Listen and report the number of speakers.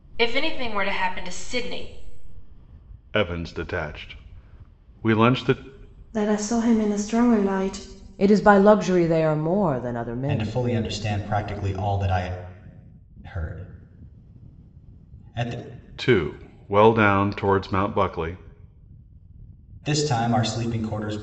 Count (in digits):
5